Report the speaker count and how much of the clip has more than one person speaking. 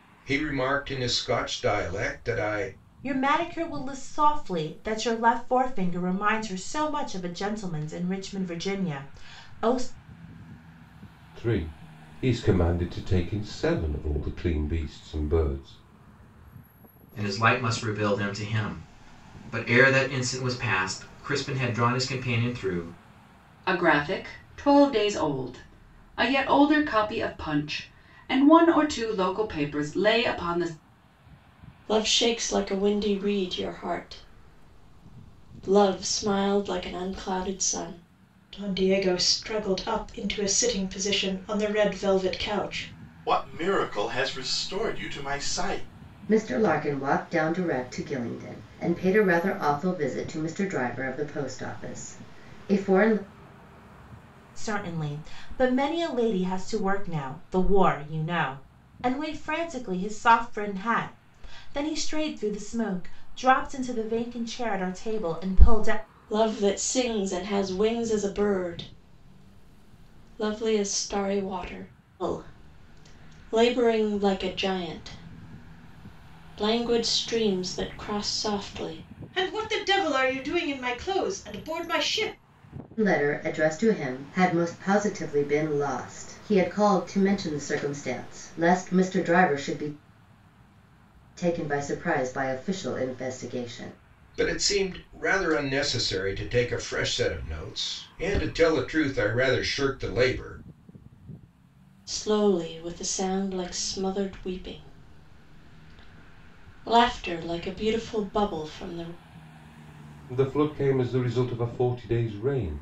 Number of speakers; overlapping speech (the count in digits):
9, no overlap